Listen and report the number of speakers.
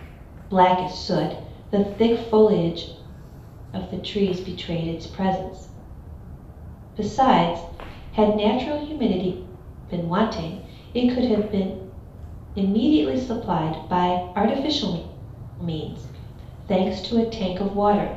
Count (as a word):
one